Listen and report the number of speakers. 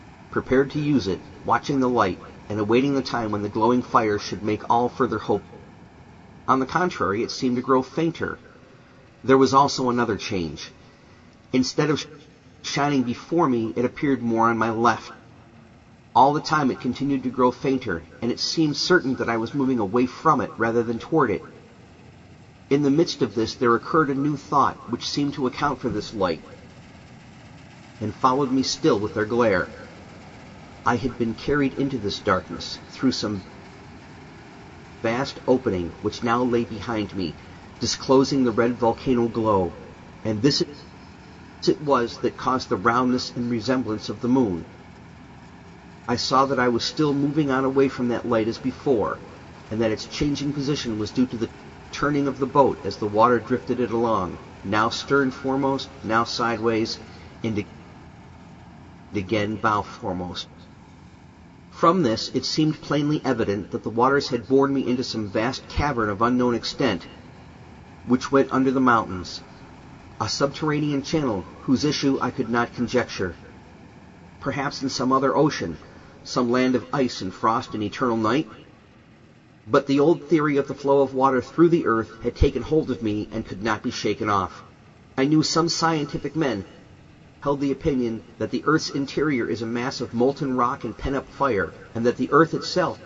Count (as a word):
one